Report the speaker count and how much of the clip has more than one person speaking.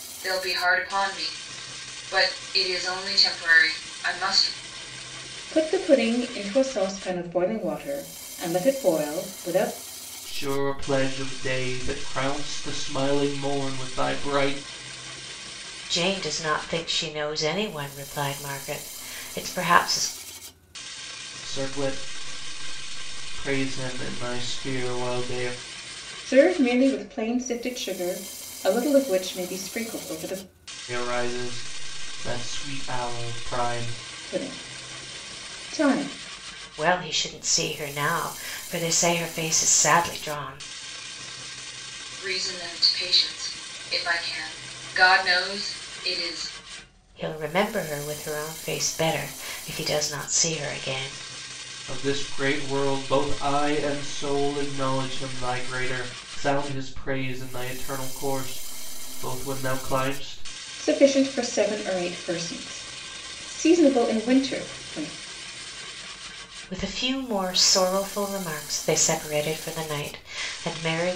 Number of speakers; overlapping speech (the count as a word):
four, no overlap